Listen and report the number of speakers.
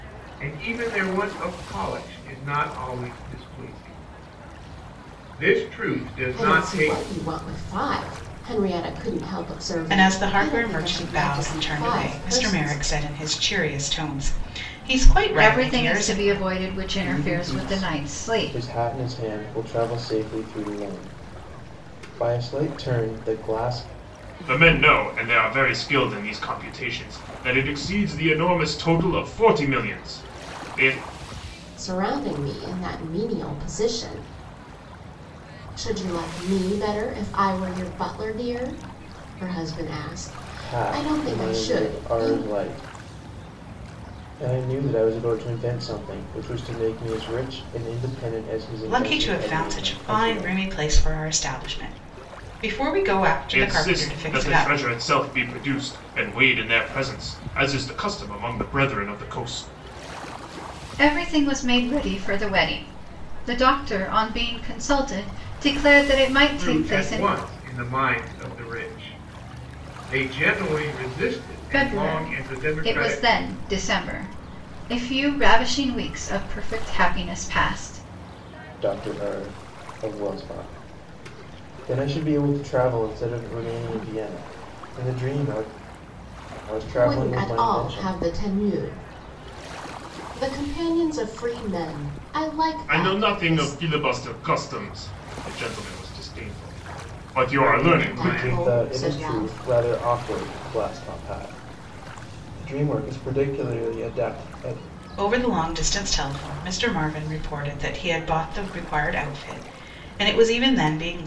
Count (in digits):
6